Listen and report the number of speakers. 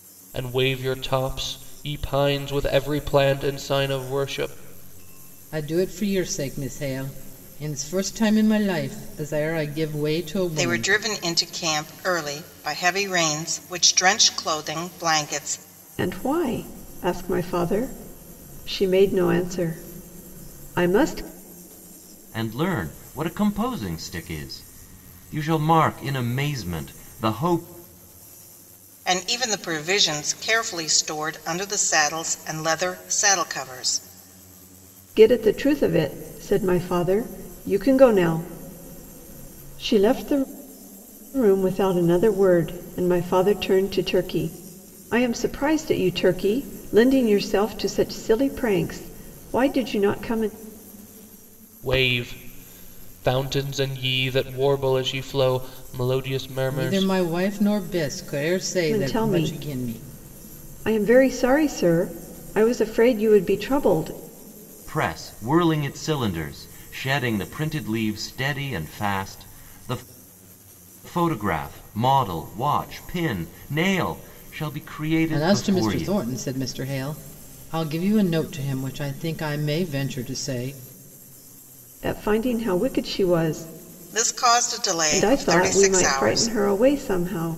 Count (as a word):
five